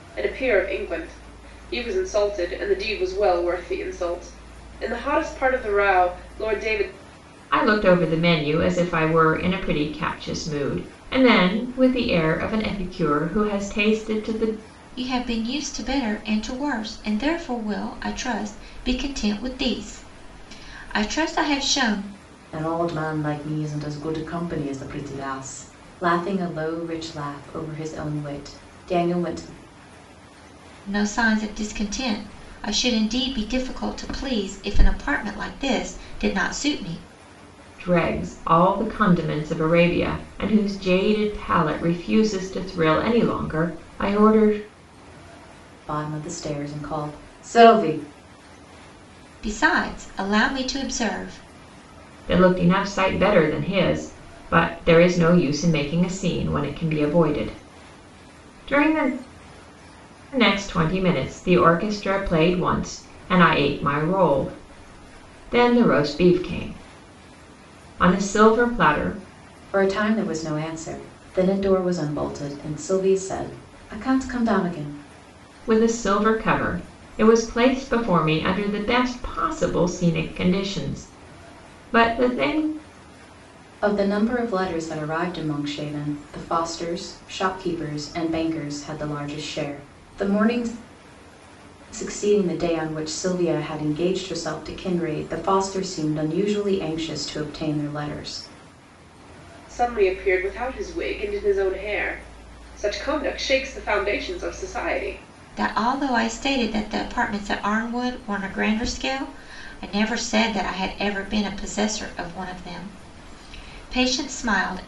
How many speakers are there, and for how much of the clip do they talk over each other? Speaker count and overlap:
four, no overlap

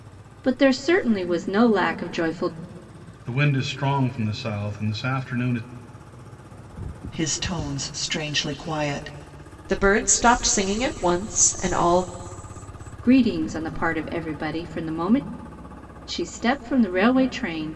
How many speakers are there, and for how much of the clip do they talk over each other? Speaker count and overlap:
four, no overlap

